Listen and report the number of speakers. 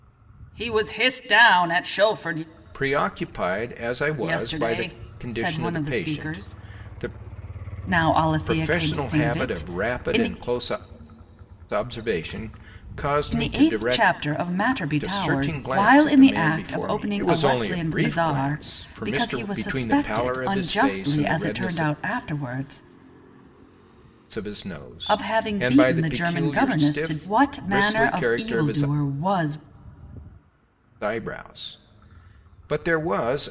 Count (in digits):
2